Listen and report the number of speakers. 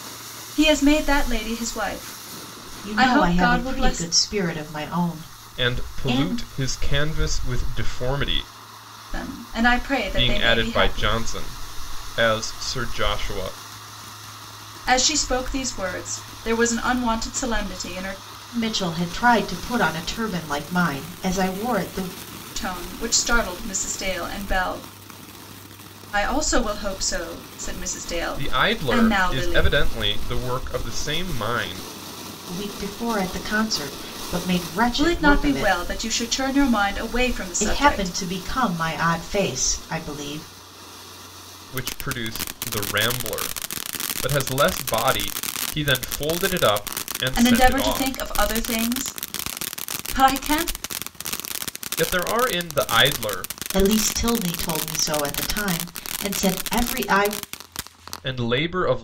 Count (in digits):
3